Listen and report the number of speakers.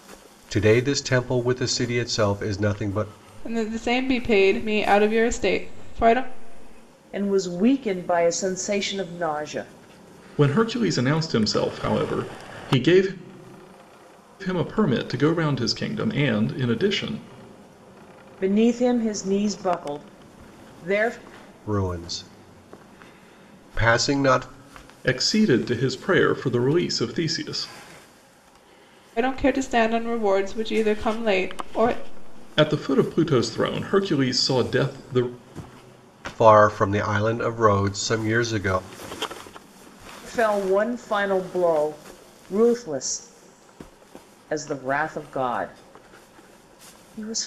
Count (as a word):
four